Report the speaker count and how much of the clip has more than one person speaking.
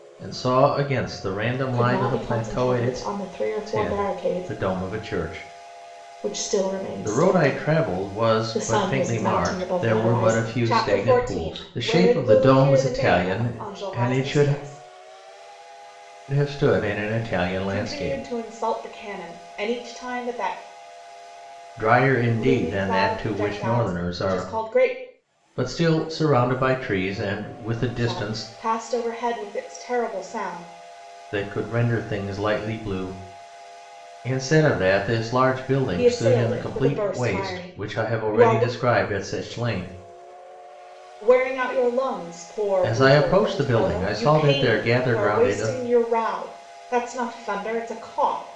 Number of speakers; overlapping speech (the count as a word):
two, about 39%